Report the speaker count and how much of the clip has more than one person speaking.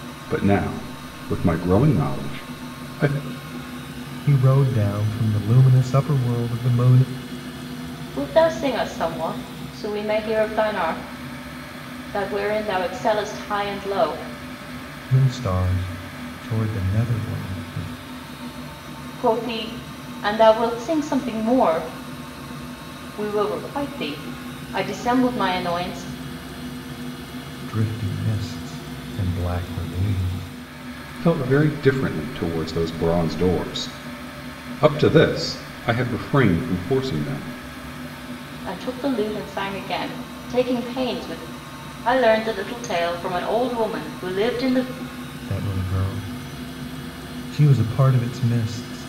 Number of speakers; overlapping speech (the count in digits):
3, no overlap